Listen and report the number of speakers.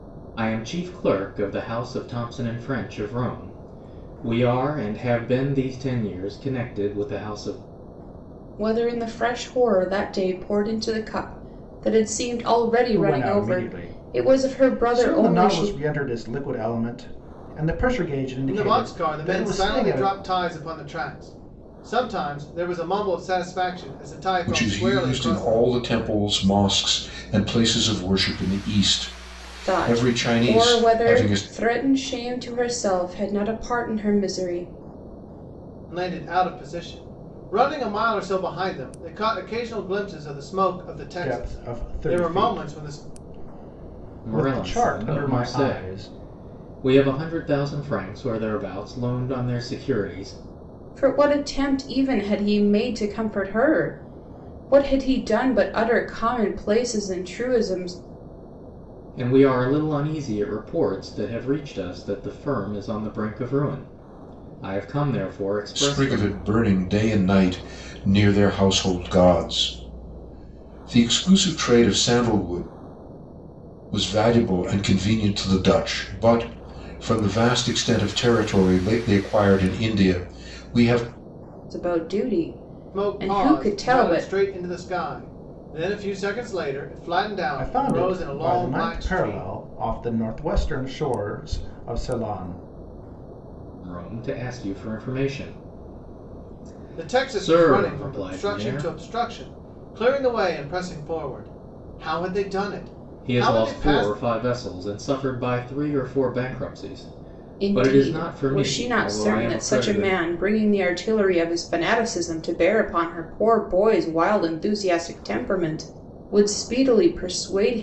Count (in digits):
5